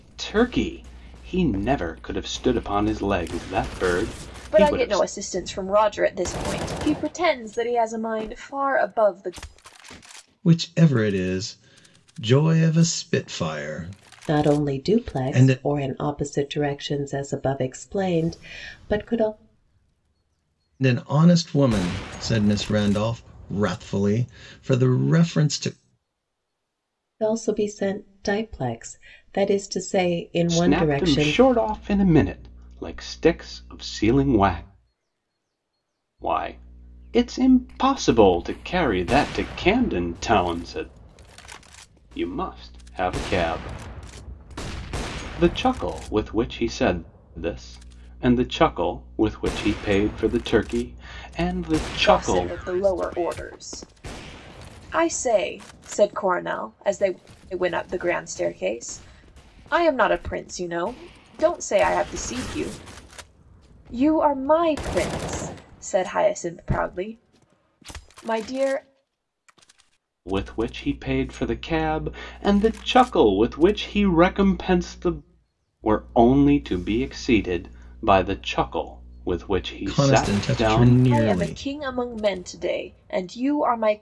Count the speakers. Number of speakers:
four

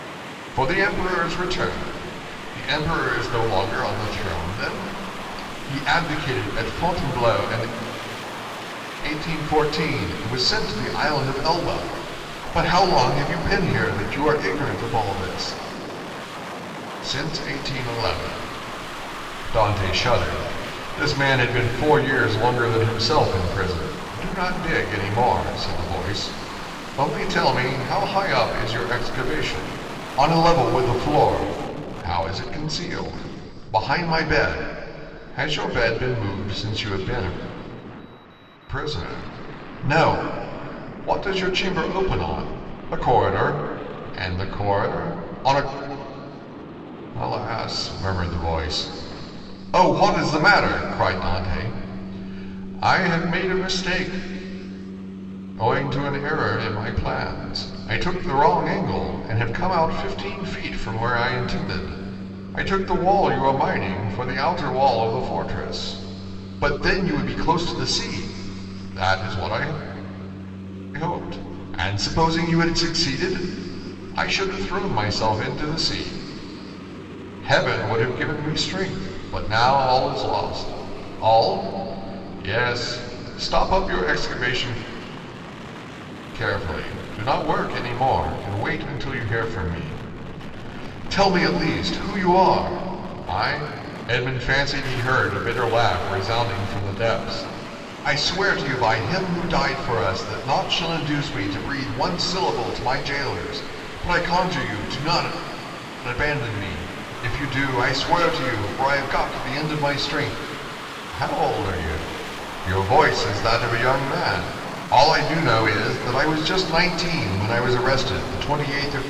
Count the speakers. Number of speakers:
one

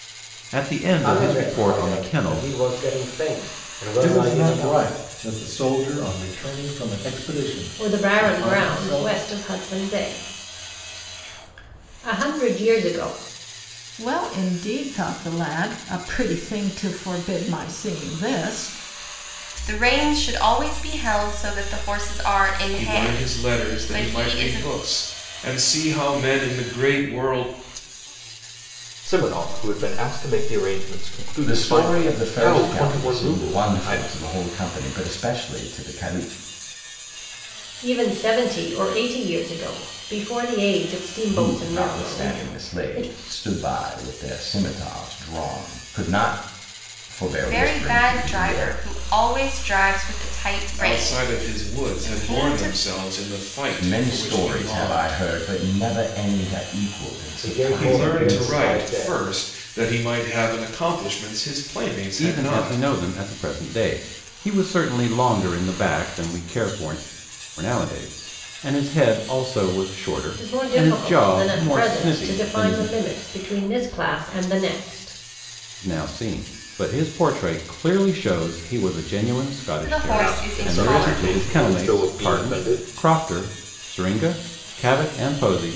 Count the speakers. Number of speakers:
nine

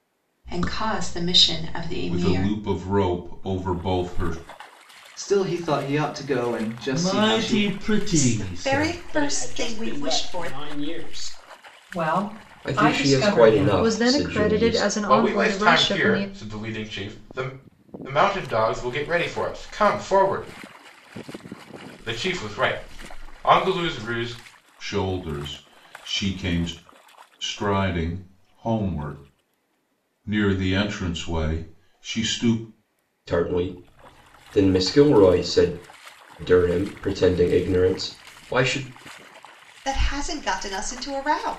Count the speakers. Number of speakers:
ten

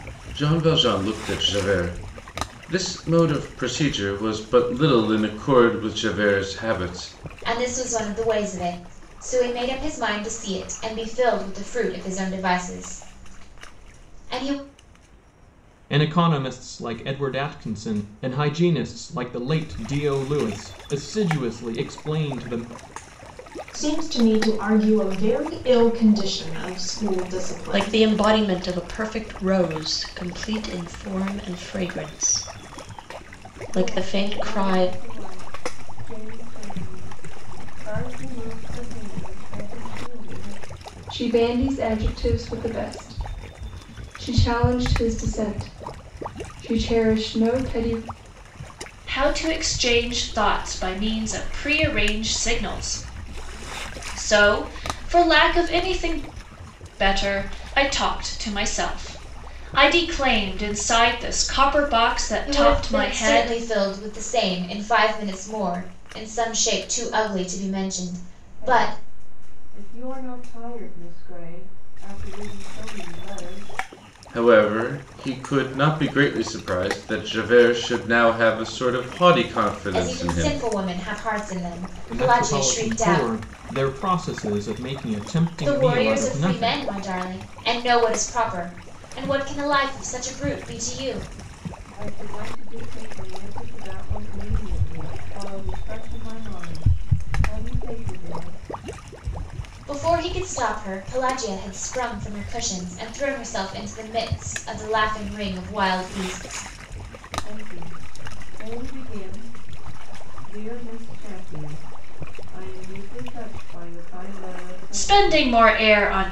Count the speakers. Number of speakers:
eight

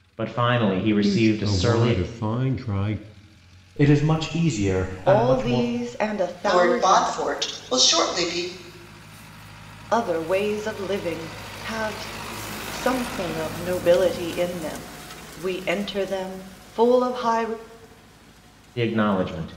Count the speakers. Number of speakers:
five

